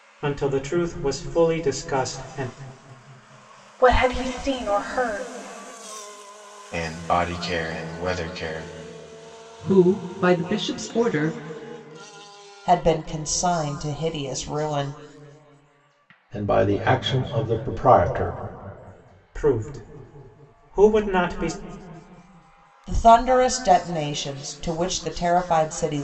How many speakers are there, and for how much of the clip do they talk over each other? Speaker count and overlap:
six, no overlap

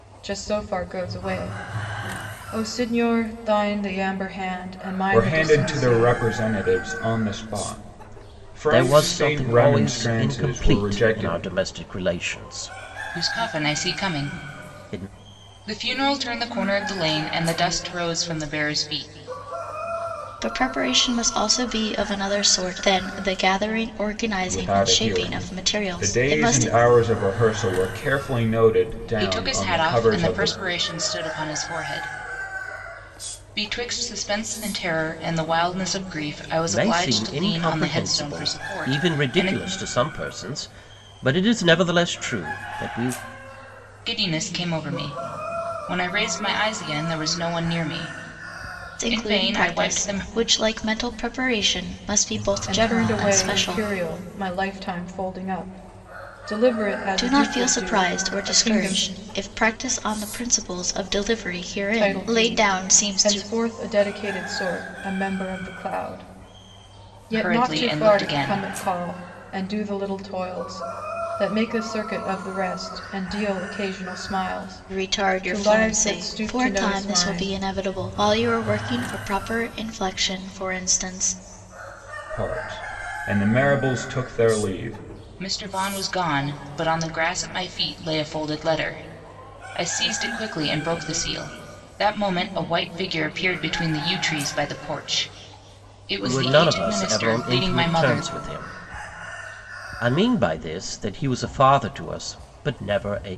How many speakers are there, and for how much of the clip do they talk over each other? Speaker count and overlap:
five, about 24%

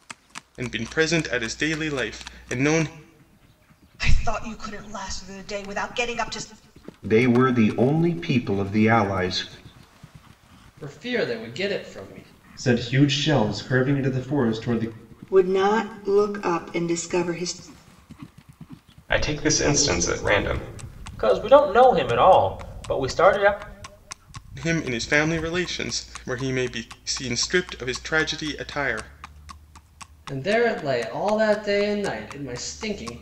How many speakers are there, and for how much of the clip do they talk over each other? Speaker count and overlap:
eight, no overlap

